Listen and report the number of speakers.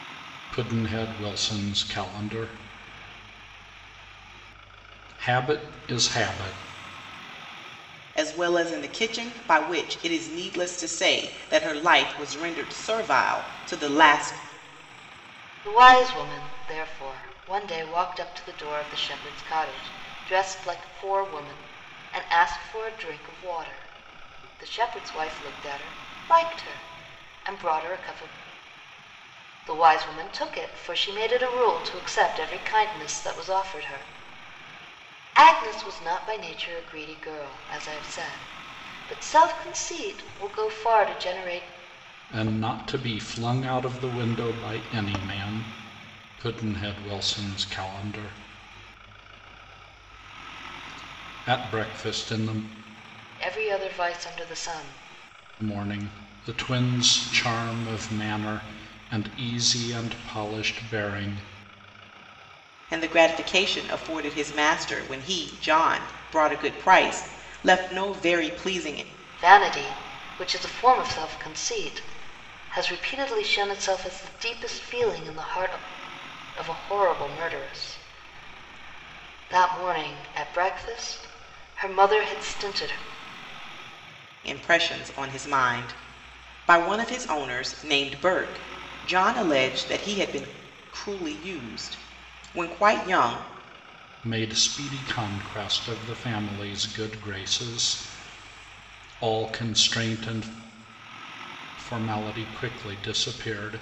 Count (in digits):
3